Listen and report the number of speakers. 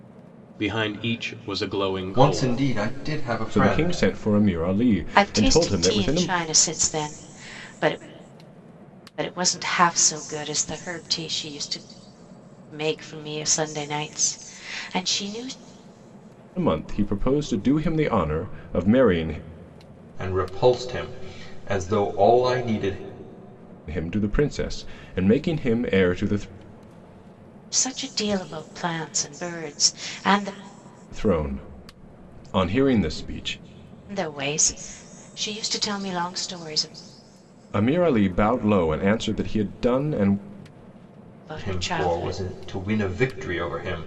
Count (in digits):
4